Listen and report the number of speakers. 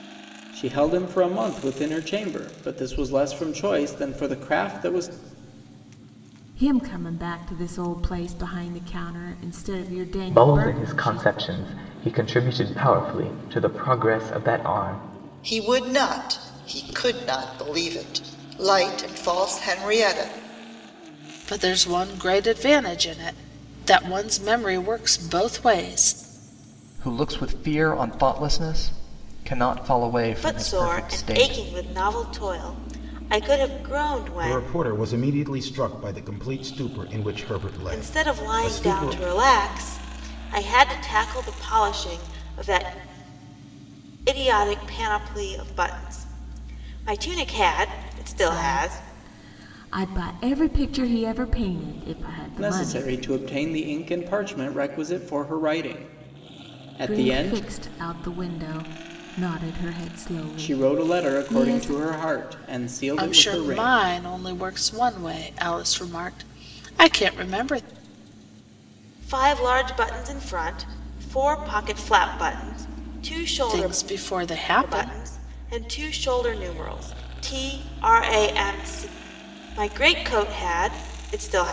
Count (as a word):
eight